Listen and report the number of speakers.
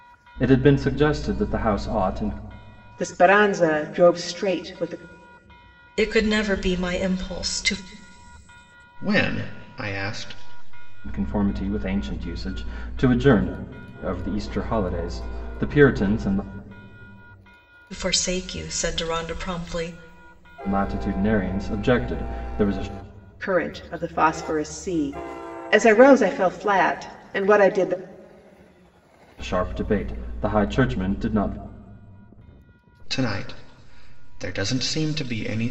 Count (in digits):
4